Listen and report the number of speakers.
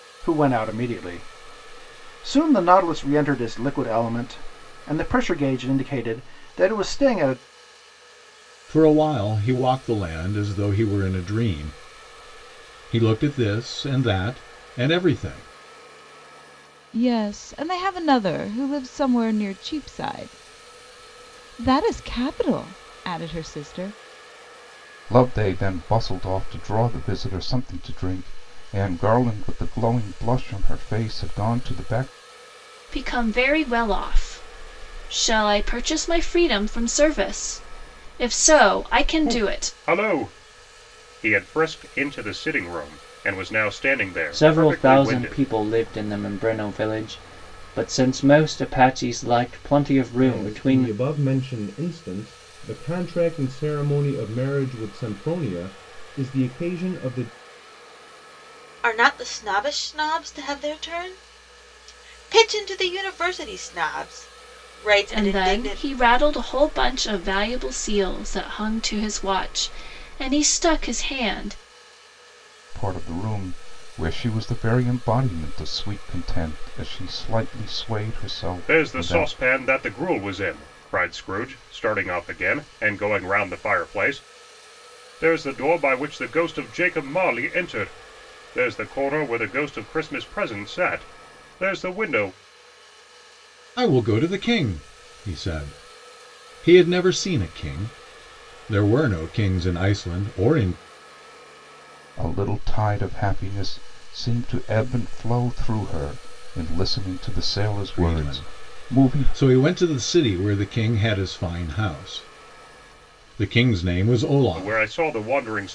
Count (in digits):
9